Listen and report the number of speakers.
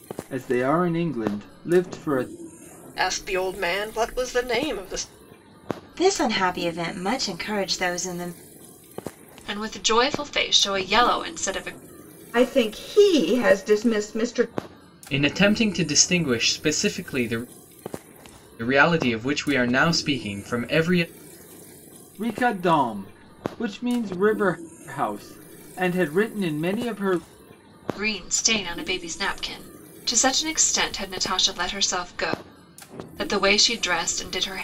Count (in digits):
6